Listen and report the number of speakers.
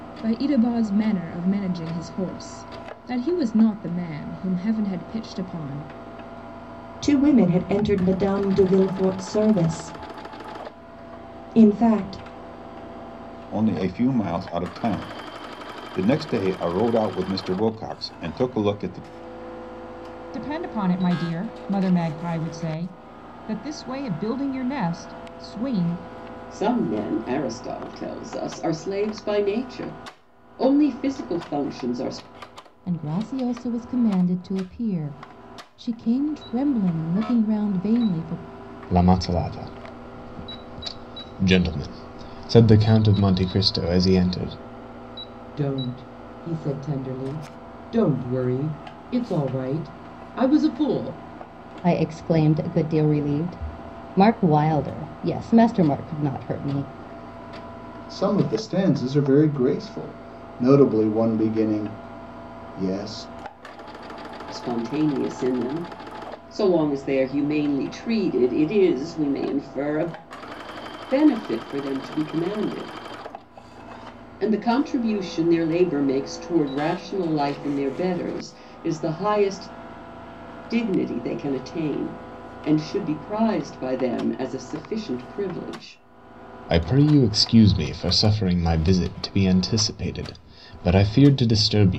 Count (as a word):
ten